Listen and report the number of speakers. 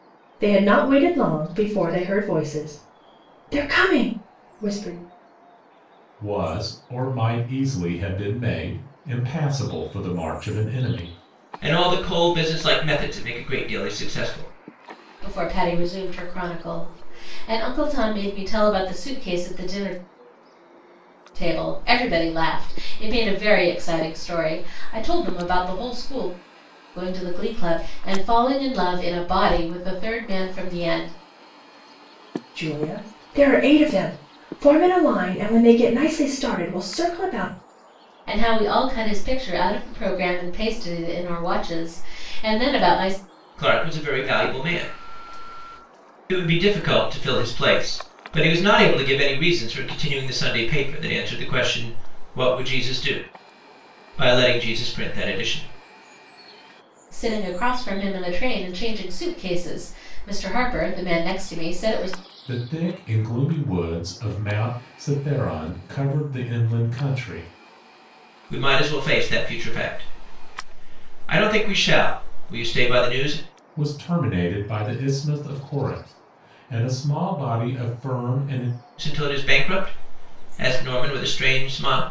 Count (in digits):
4